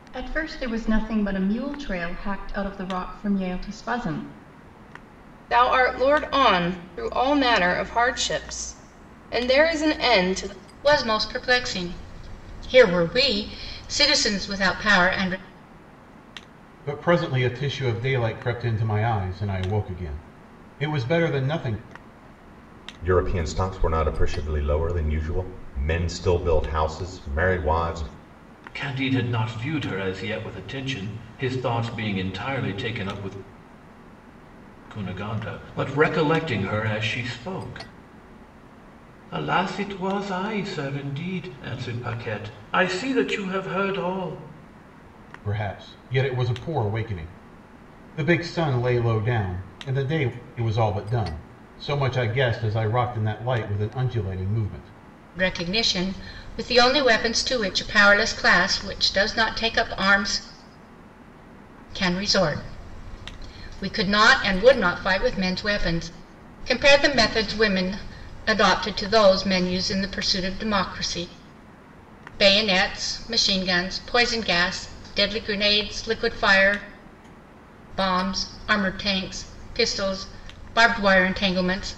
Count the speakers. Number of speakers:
six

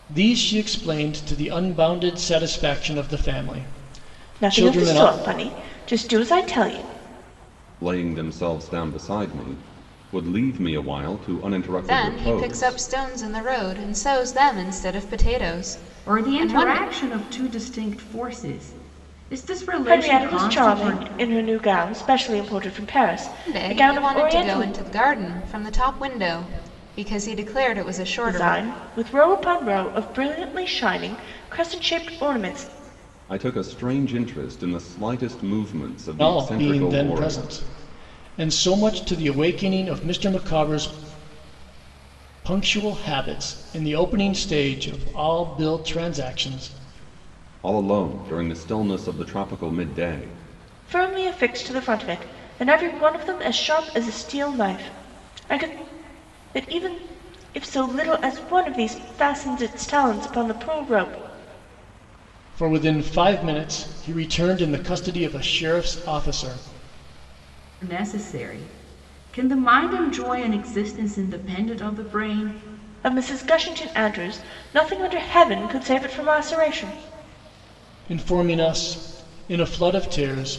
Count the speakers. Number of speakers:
five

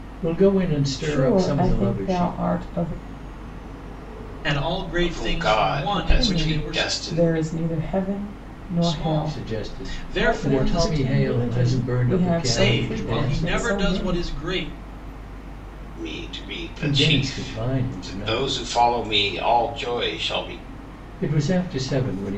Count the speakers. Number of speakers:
four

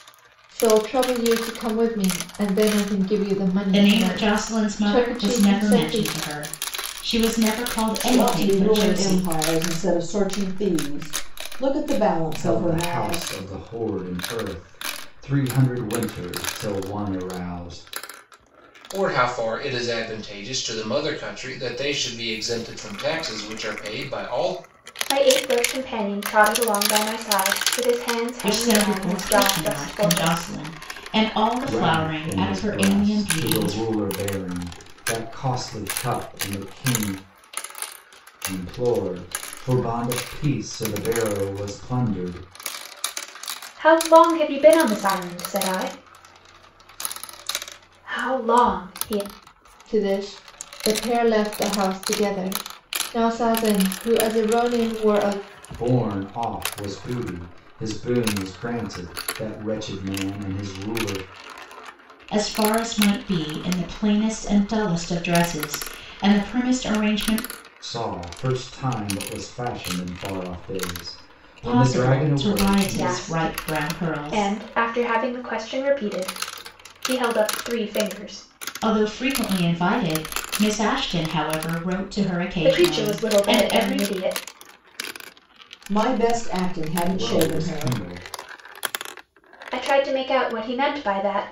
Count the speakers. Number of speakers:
six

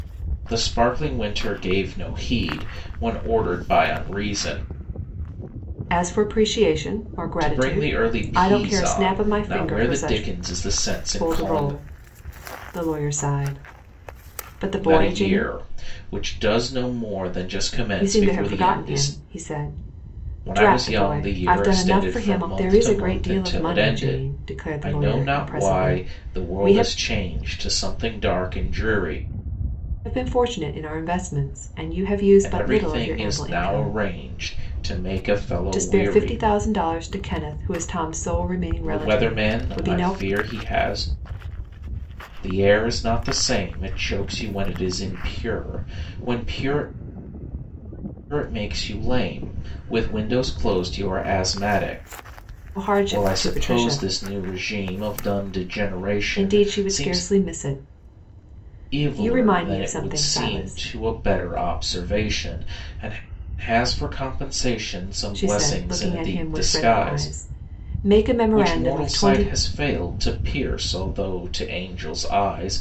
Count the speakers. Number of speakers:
two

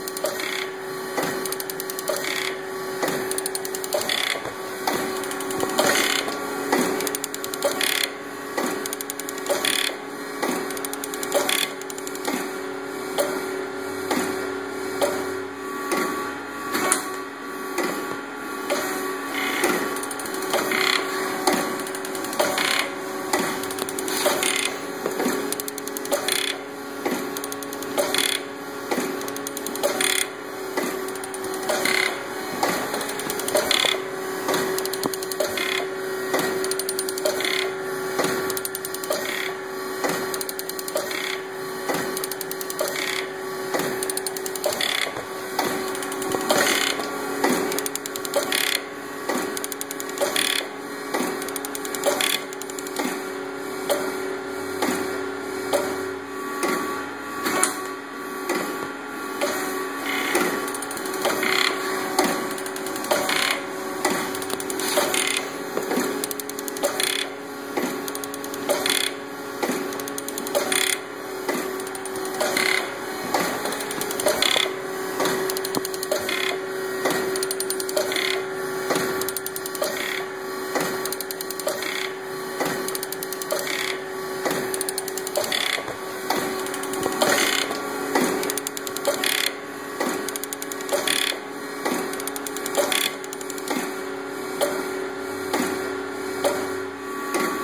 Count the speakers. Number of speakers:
zero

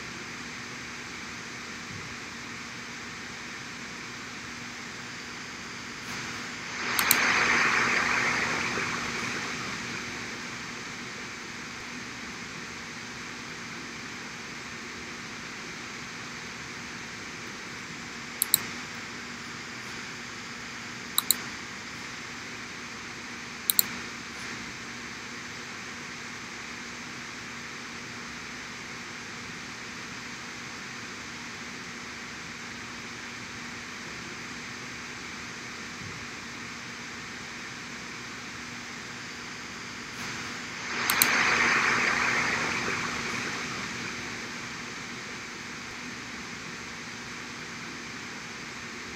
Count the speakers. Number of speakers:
zero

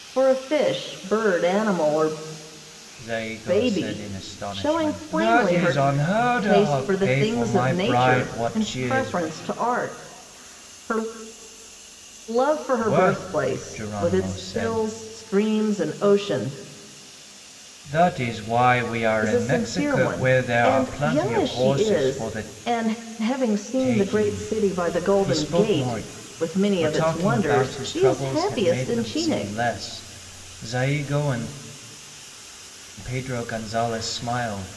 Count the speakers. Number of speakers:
two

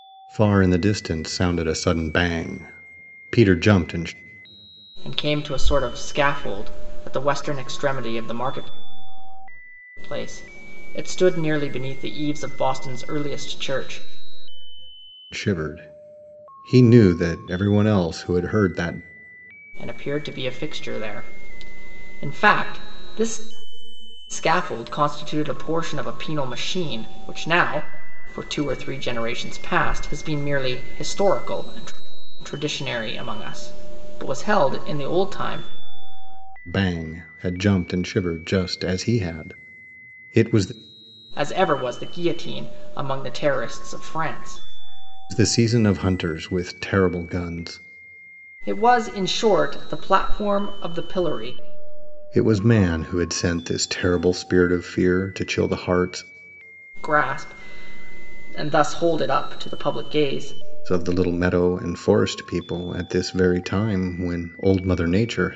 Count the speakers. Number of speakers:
two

